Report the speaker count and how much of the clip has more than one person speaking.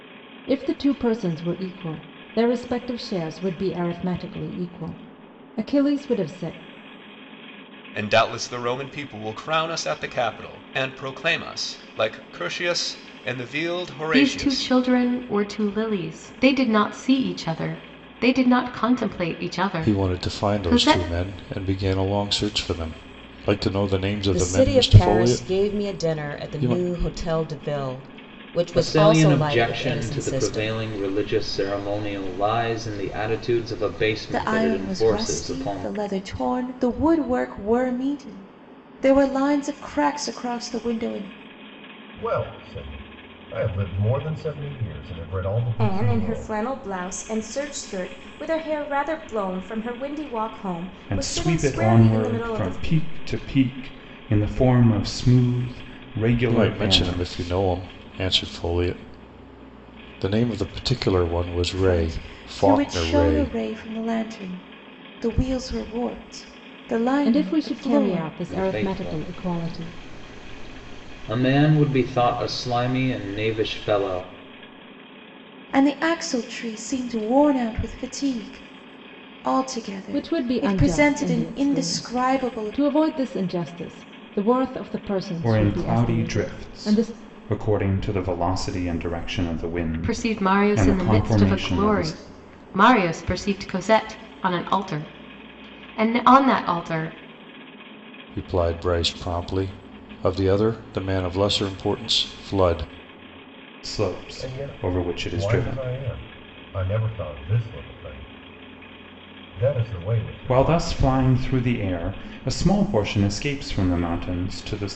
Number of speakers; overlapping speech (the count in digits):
10, about 22%